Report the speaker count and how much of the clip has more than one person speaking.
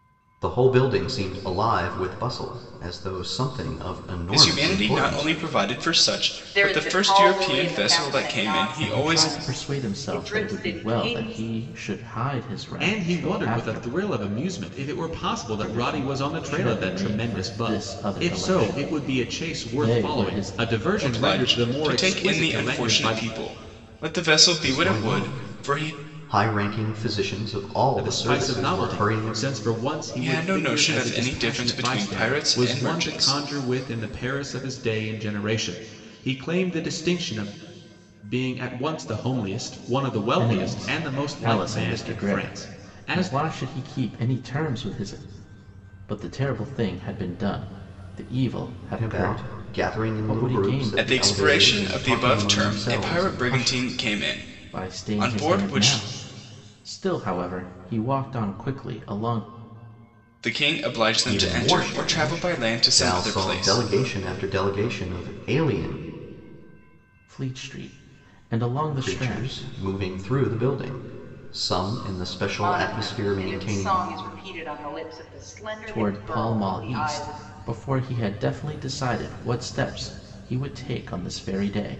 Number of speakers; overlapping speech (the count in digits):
5, about 44%